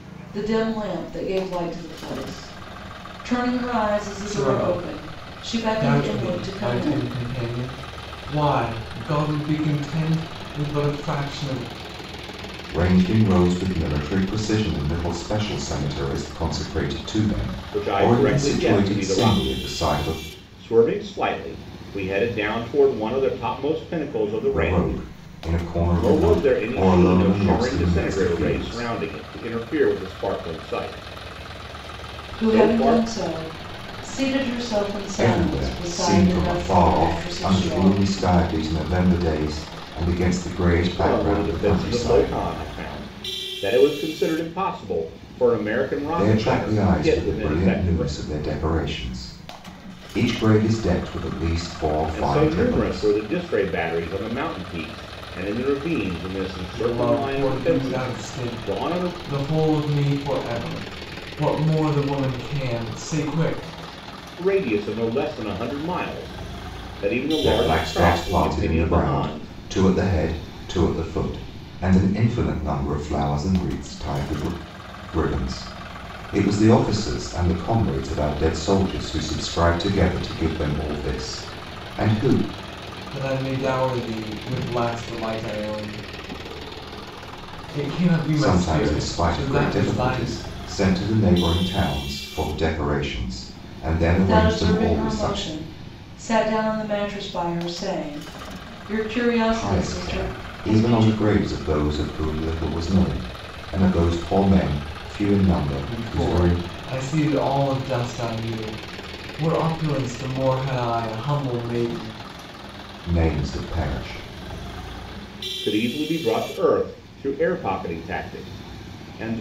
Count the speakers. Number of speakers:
4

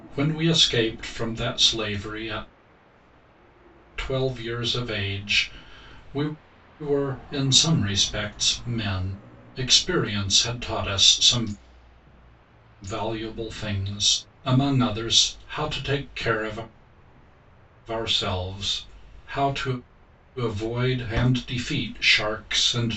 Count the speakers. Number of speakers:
1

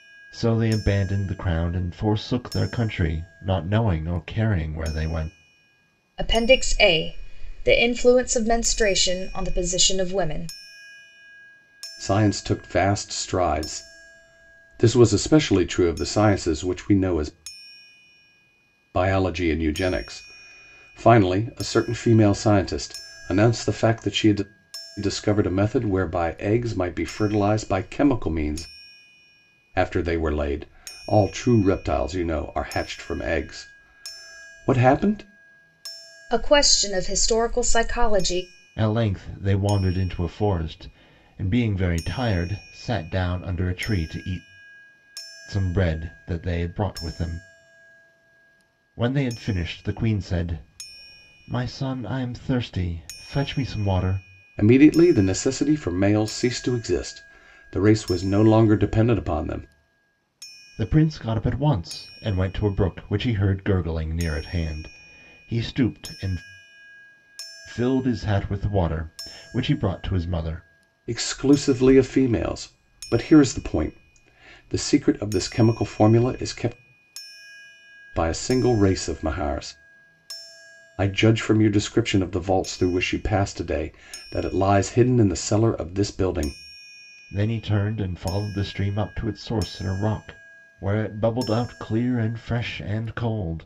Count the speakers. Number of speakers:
3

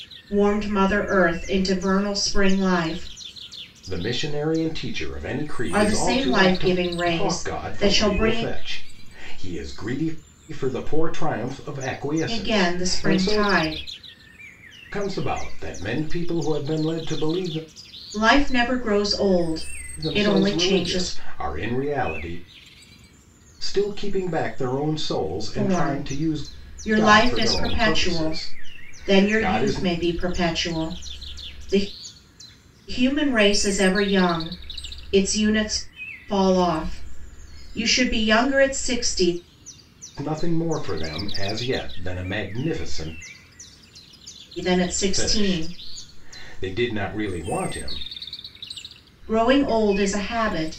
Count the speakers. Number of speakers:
2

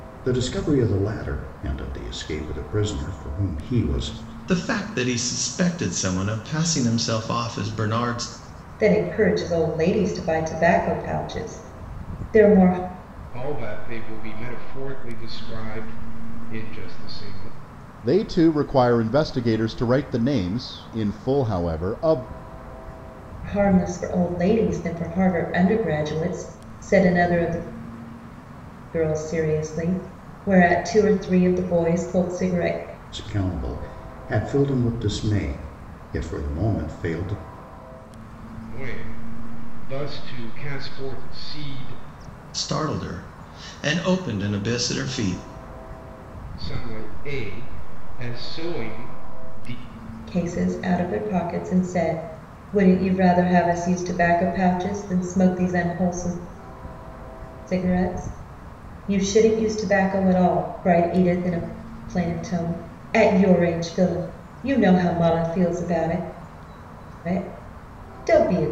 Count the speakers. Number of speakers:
5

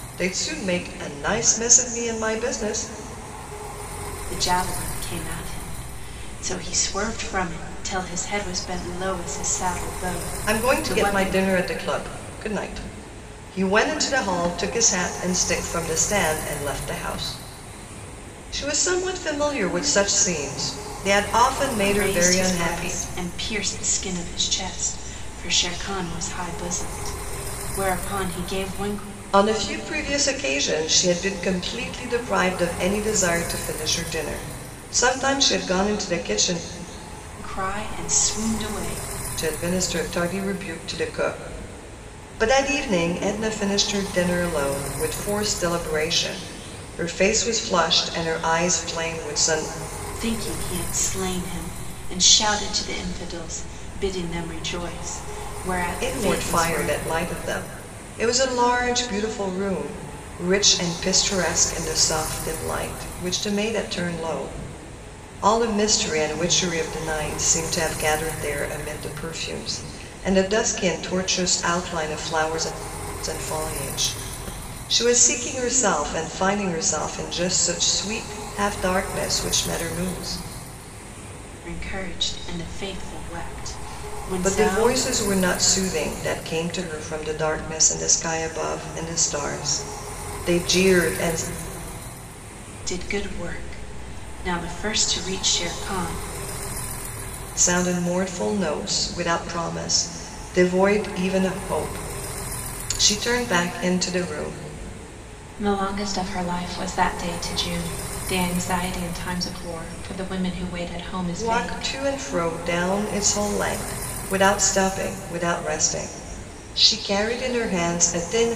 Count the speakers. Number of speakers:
2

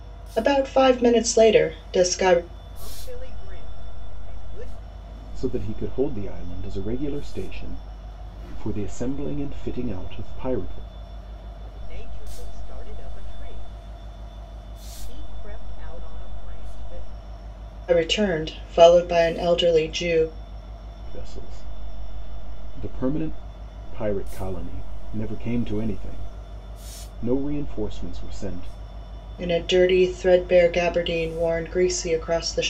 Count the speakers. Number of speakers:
3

